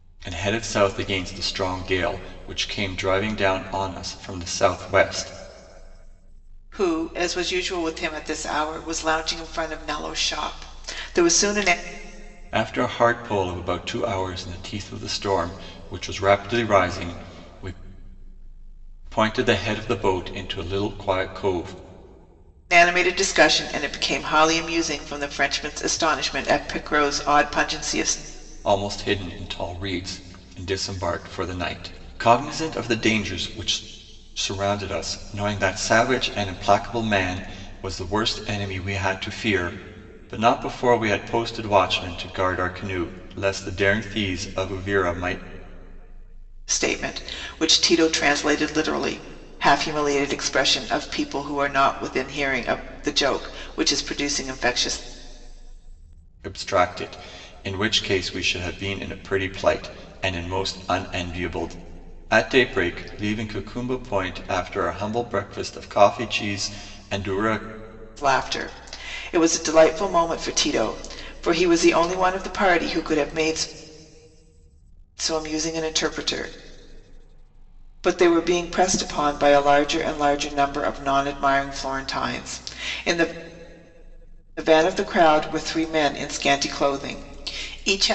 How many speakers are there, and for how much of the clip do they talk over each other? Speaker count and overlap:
2, no overlap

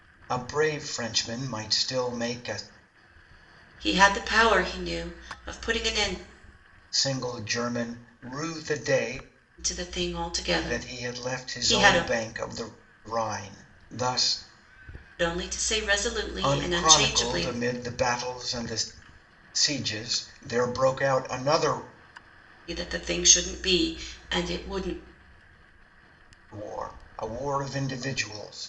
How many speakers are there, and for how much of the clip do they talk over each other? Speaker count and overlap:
2, about 9%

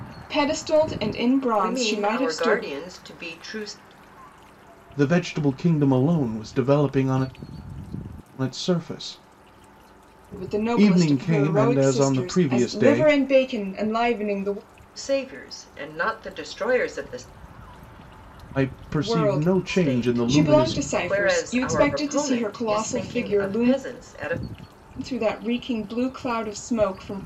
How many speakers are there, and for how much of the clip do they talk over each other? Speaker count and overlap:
3, about 30%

